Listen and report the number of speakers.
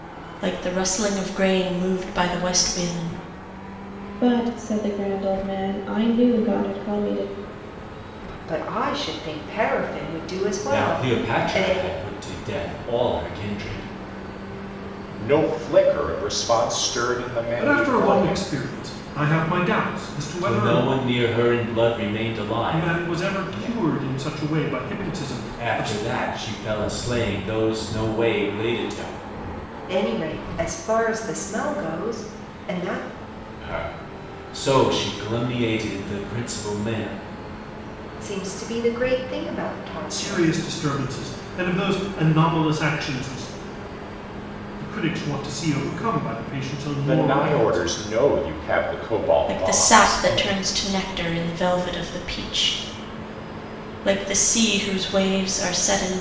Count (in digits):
6